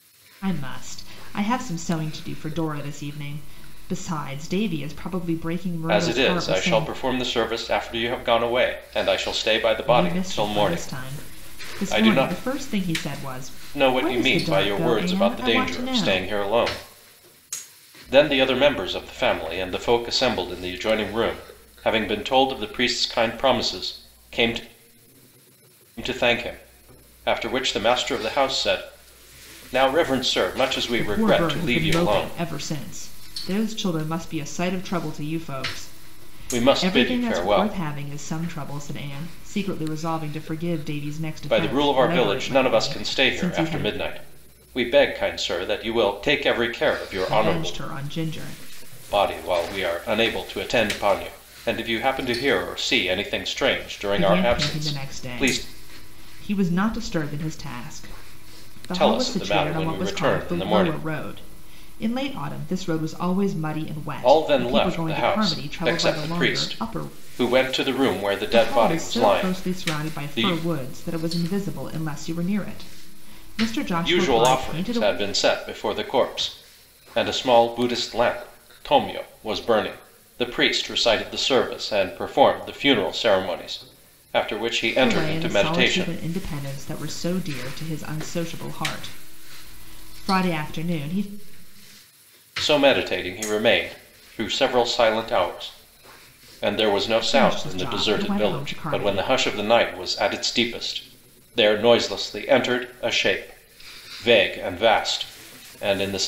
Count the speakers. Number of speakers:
2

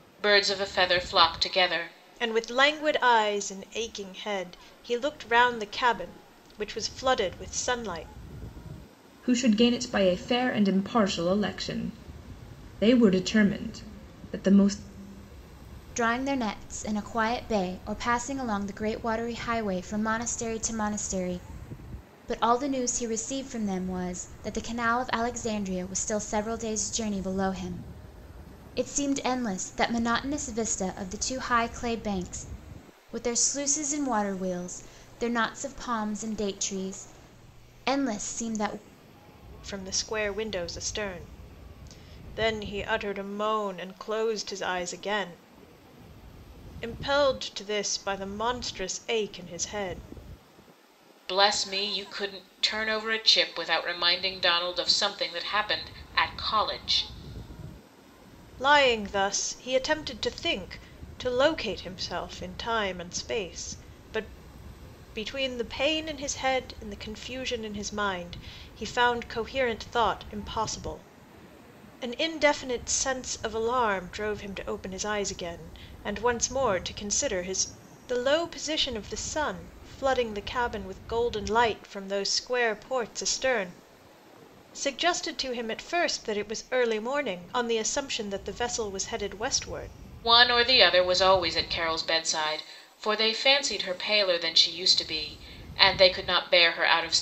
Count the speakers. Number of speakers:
4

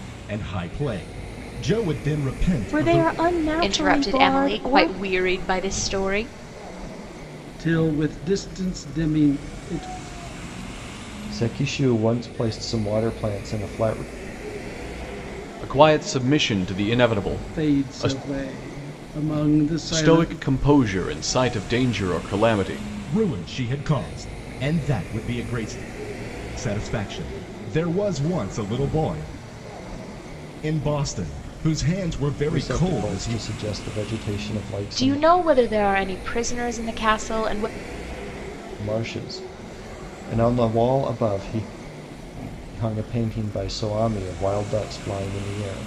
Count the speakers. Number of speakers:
6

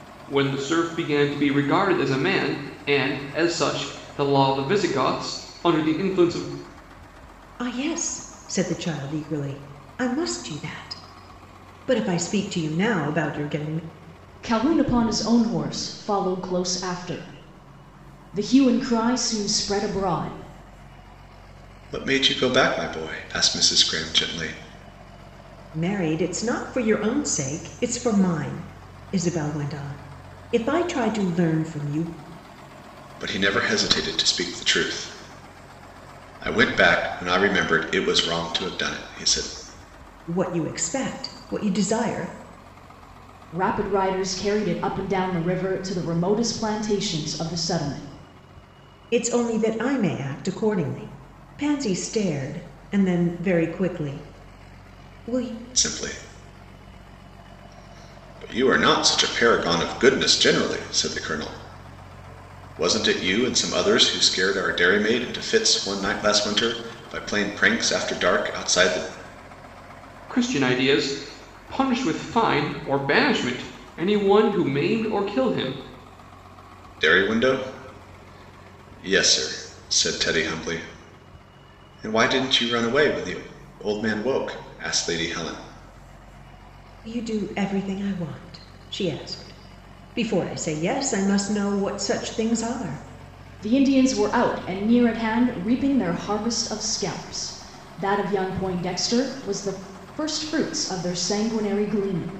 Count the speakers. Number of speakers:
4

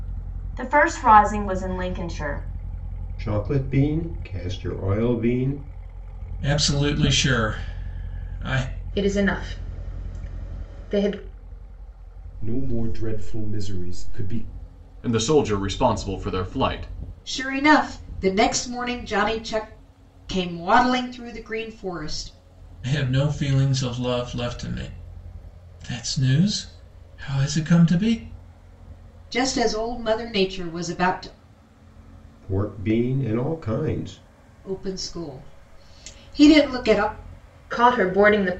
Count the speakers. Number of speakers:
7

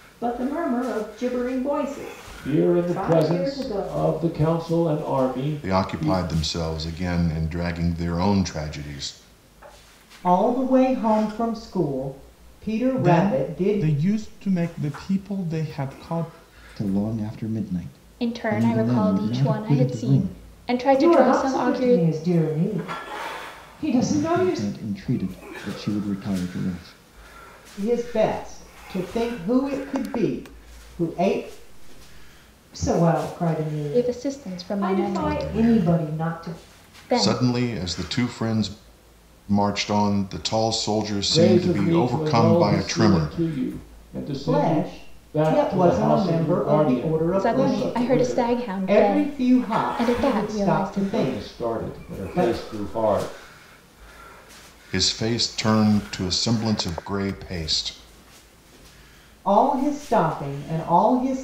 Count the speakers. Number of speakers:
8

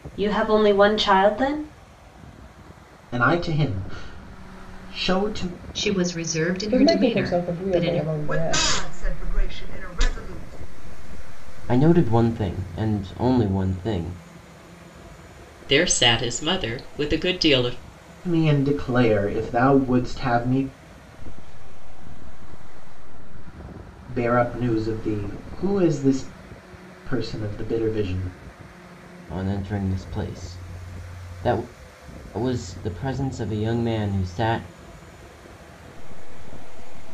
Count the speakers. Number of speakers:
8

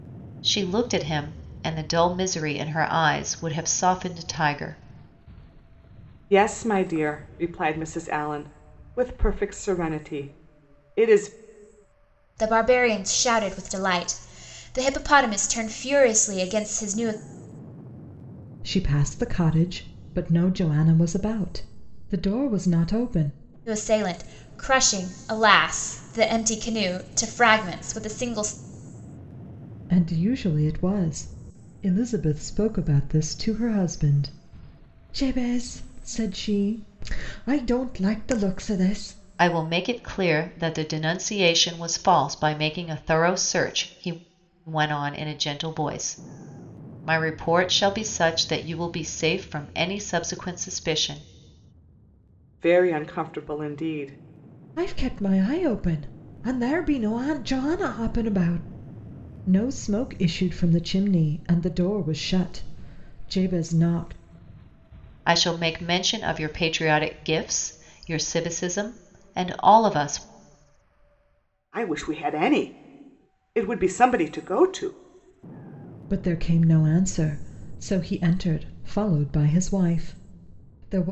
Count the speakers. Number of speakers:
4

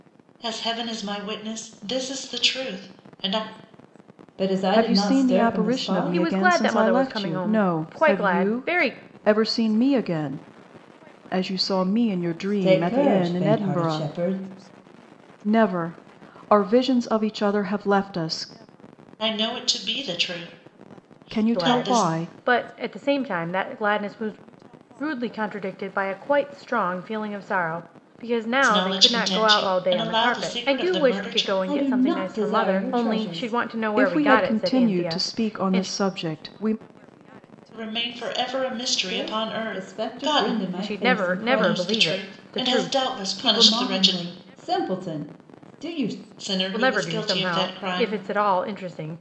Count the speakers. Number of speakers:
4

